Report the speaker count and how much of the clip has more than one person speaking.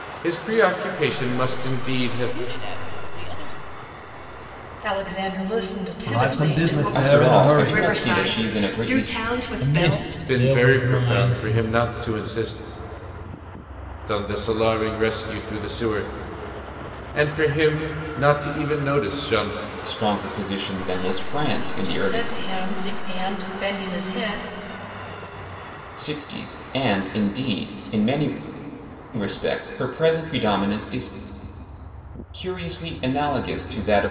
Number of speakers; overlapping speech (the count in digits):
7, about 26%